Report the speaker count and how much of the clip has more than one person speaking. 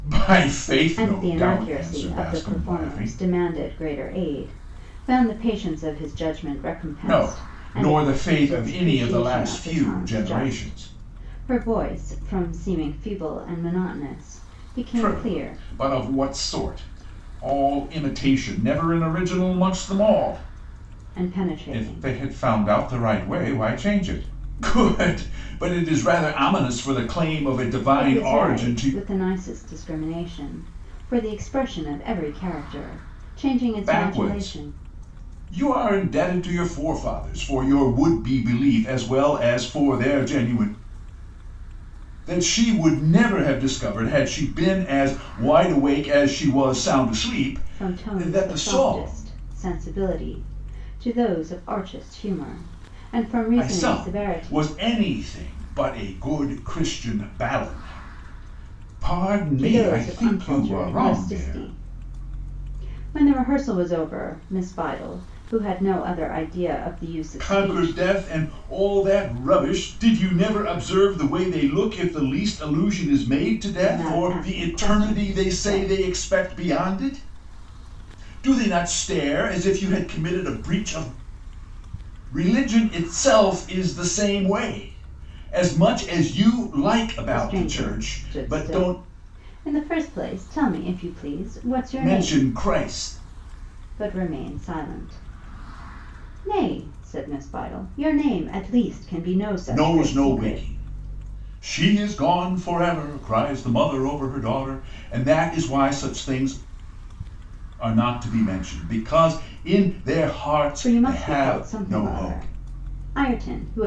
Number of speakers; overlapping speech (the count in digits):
2, about 20%